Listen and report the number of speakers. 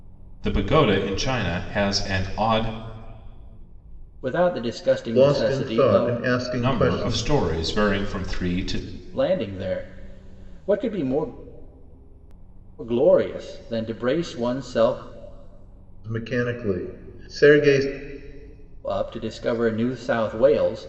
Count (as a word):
three